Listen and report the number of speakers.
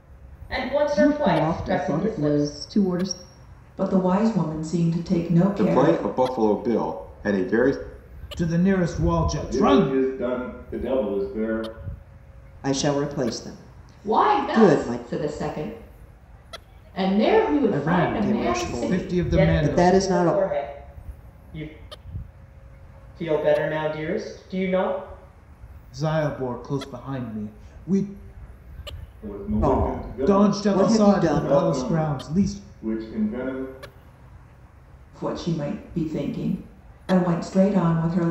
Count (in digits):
8